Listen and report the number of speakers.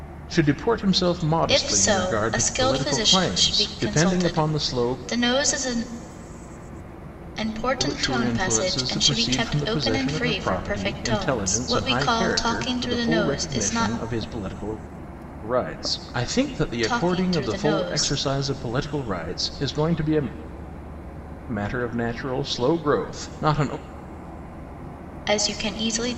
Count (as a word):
two